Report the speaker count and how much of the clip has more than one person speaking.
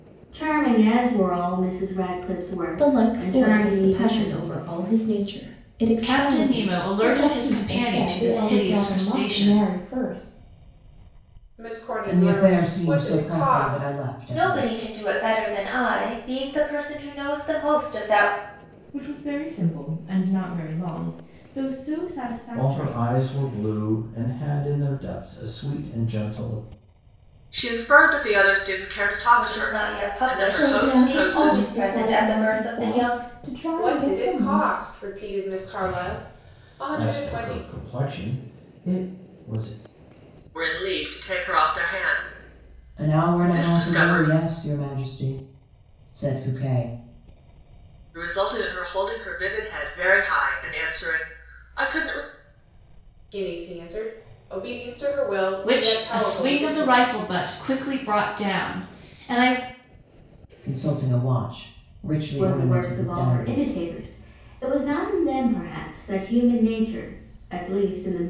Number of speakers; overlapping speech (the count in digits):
10, about 29%